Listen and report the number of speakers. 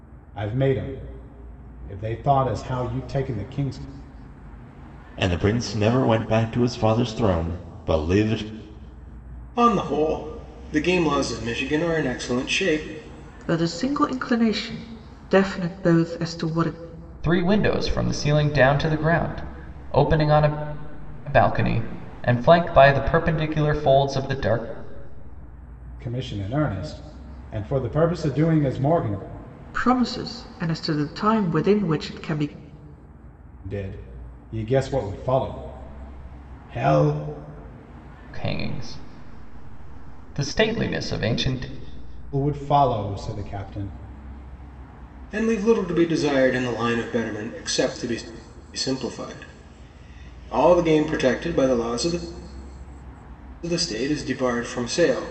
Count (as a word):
five